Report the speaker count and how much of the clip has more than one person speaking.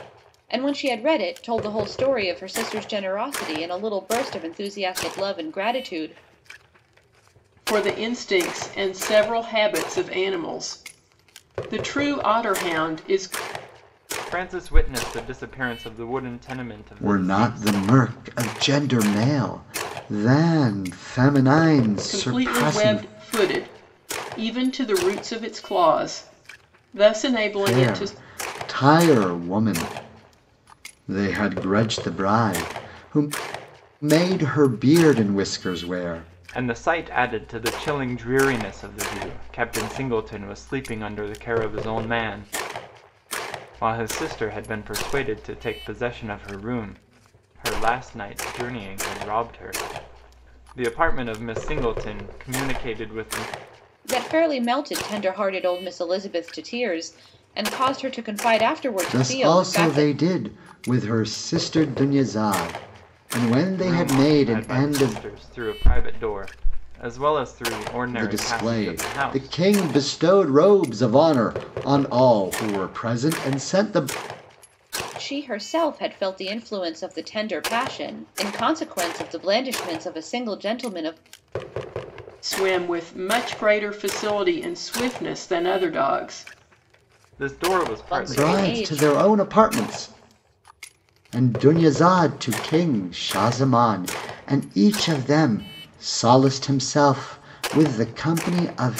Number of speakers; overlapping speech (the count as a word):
four, about 8%